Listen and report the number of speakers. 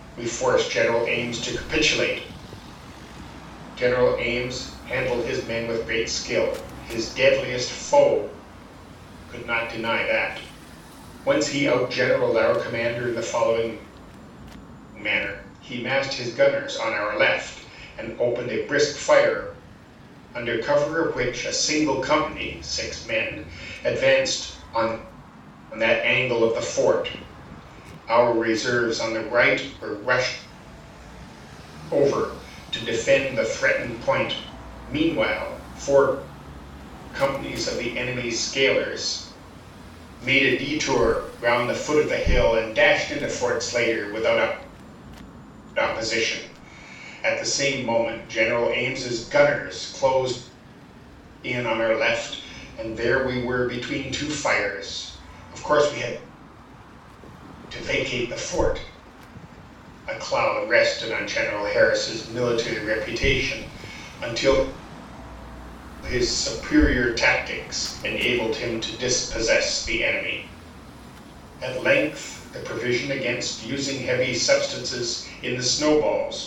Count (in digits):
1